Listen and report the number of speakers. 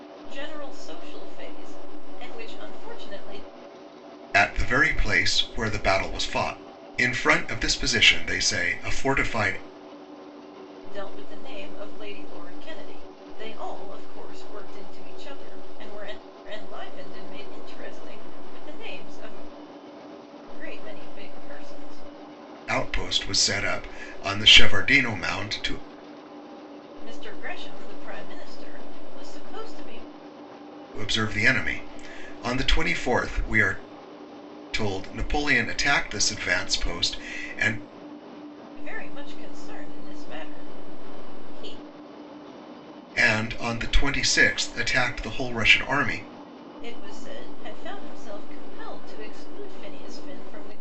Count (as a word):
two